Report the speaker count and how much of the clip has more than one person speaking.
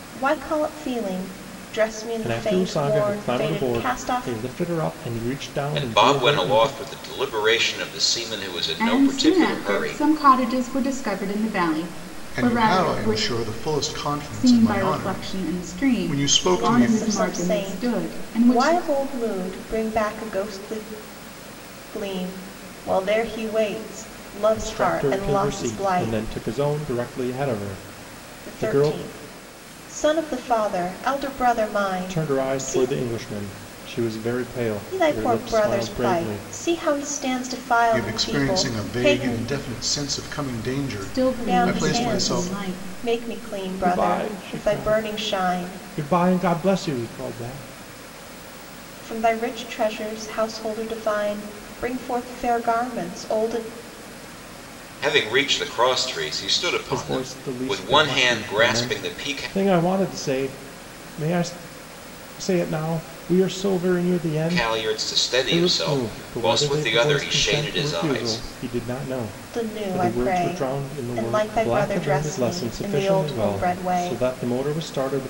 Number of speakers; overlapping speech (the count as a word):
five, about 42%